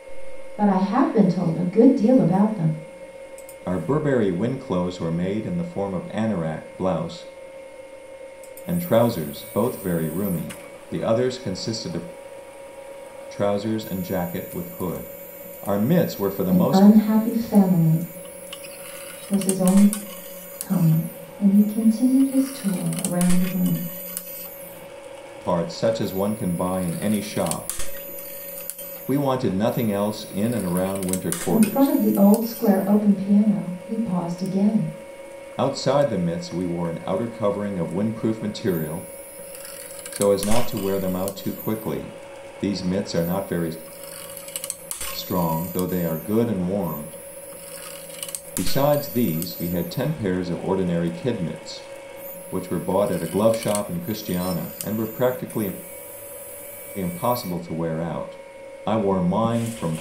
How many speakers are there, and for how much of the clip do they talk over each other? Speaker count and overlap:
two, about 2%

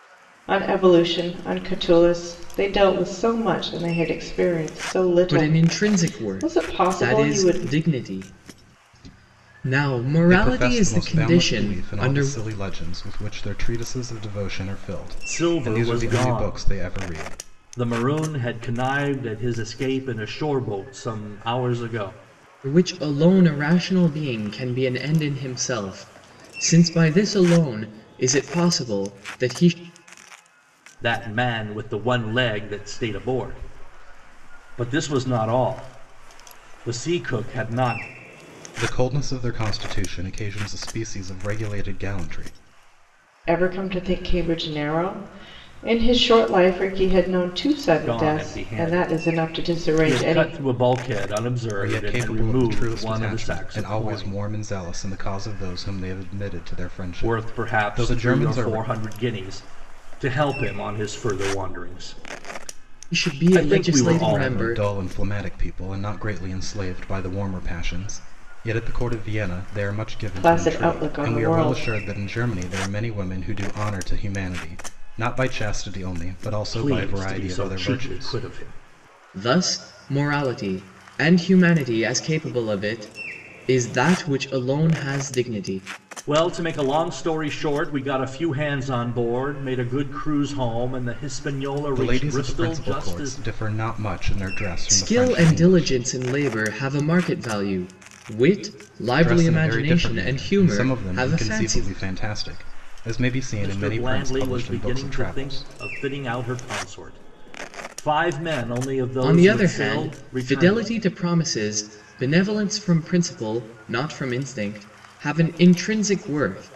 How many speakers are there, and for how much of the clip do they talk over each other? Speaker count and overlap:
four, about 24%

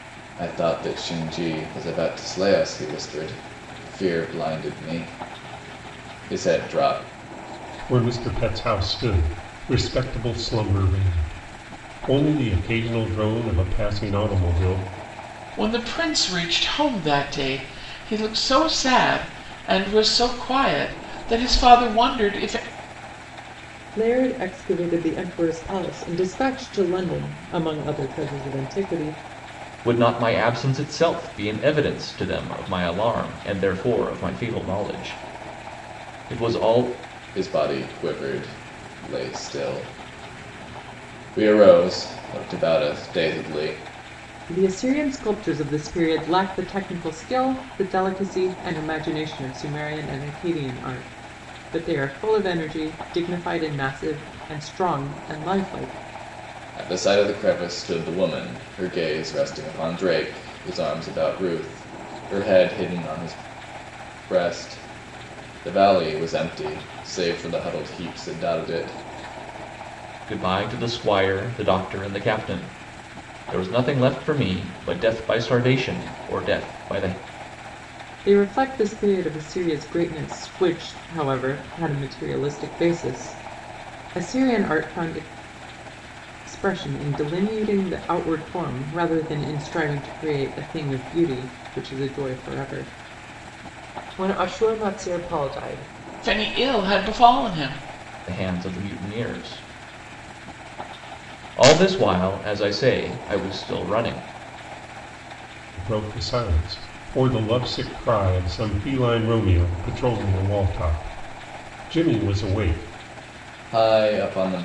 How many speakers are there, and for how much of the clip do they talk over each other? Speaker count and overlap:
five, no overlap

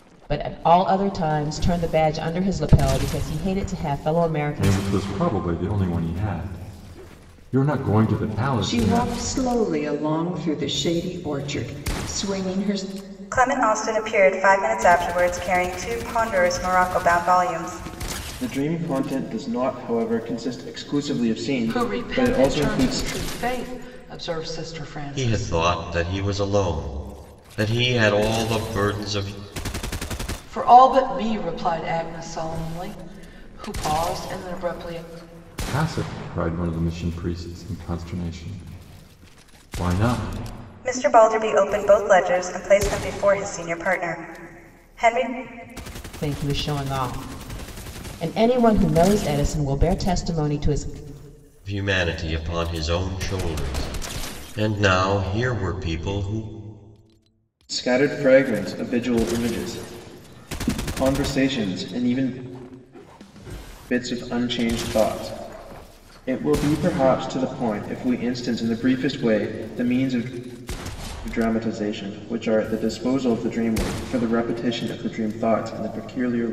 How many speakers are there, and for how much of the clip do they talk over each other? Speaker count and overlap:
seven, about 4%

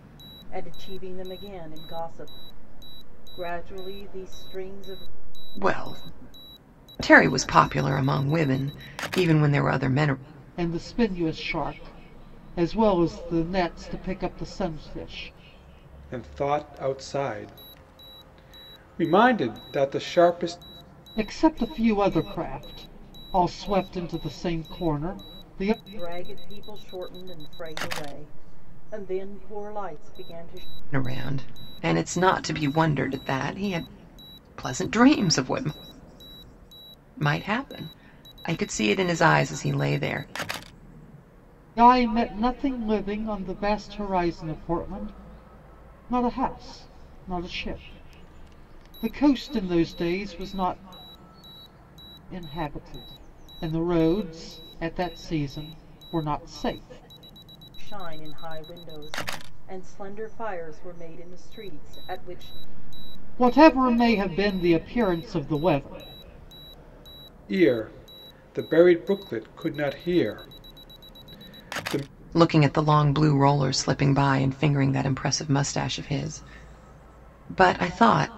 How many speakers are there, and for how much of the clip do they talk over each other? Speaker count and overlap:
four, no overlap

